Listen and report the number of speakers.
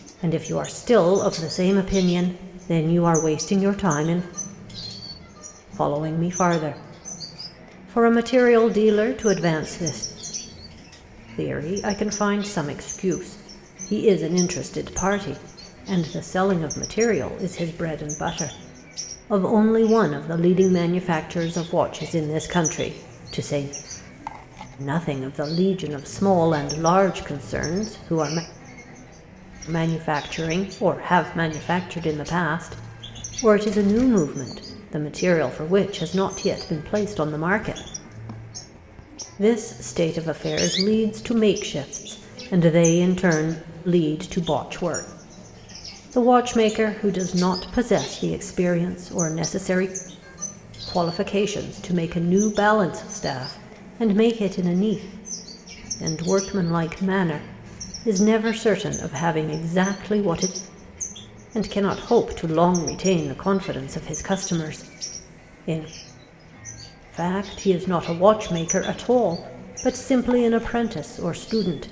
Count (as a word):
one